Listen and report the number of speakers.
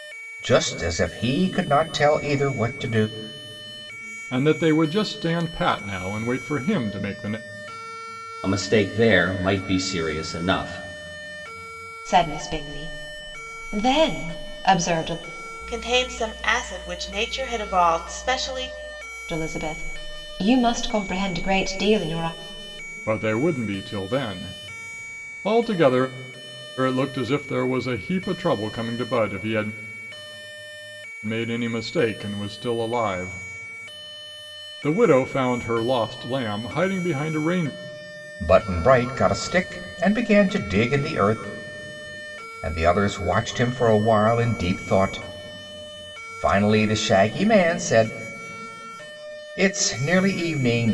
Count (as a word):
five